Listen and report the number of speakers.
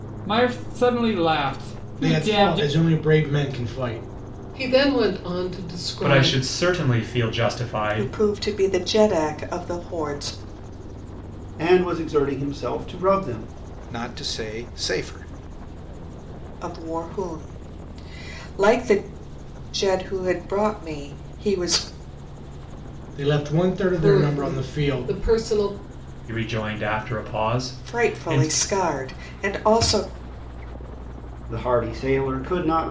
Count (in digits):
7